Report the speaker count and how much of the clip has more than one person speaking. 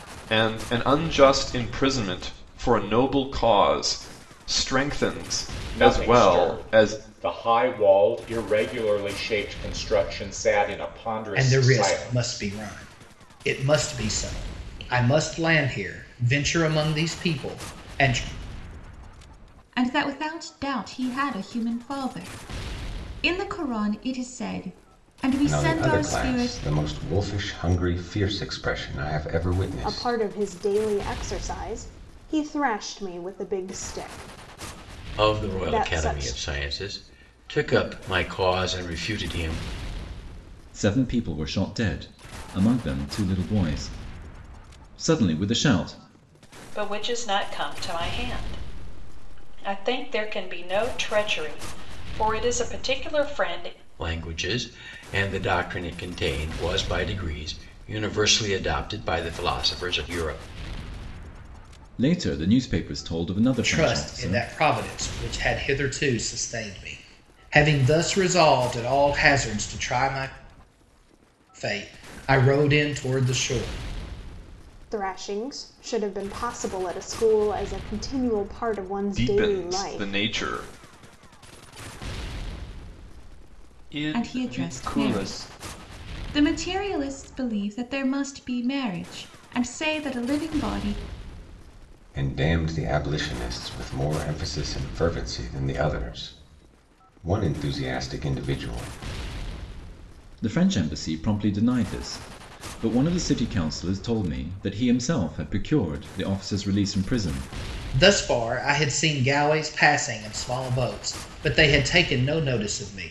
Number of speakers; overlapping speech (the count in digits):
9, about 8%